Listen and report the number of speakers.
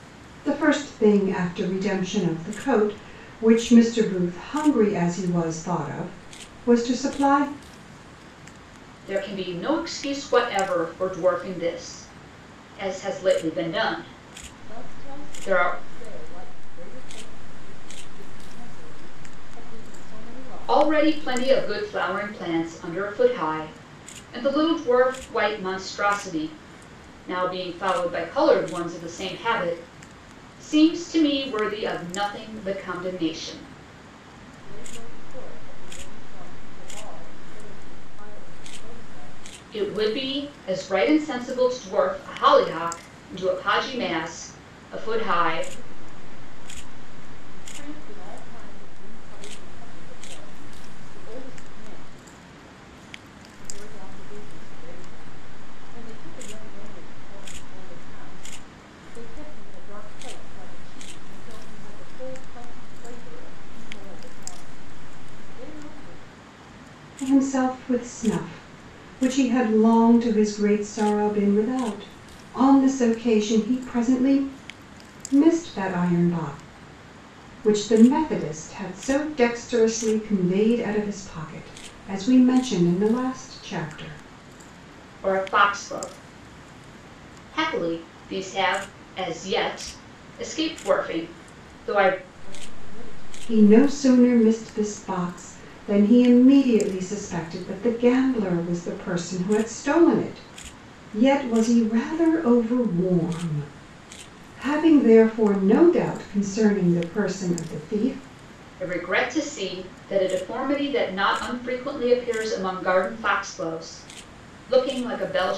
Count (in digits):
3